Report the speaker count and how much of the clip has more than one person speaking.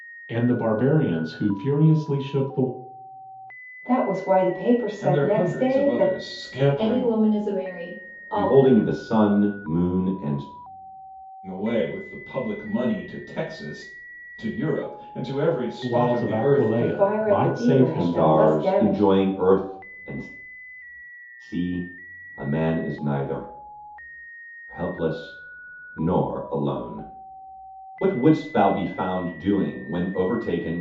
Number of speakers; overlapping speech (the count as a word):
five, about 18%